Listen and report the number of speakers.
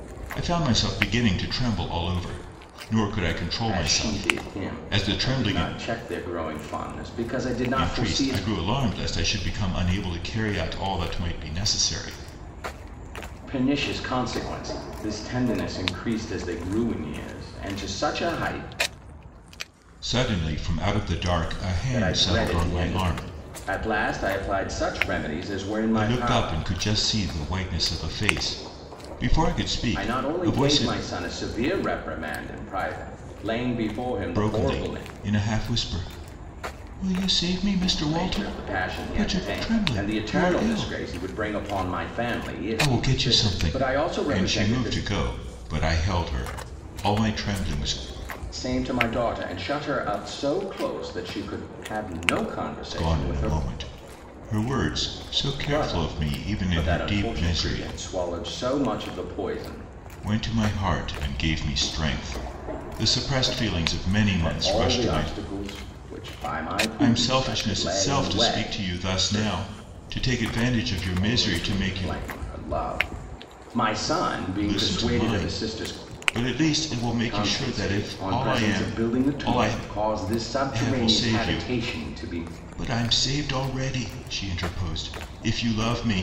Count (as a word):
two